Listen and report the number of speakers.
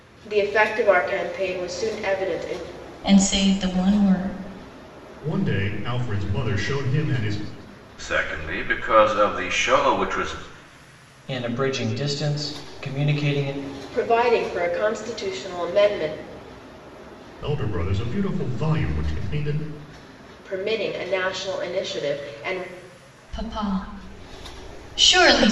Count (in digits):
5